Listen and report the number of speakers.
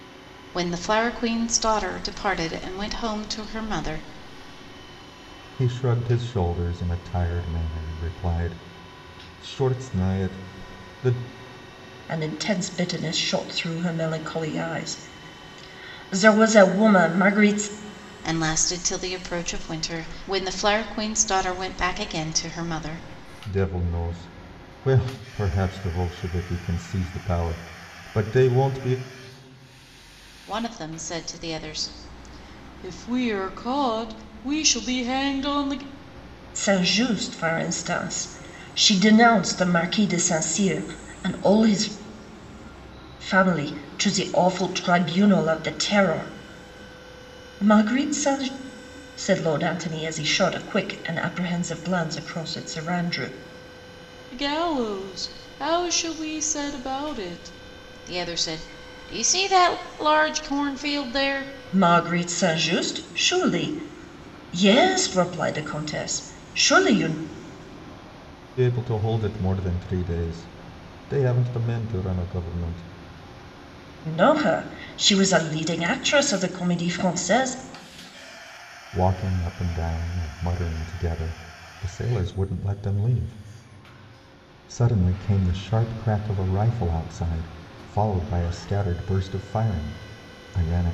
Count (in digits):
3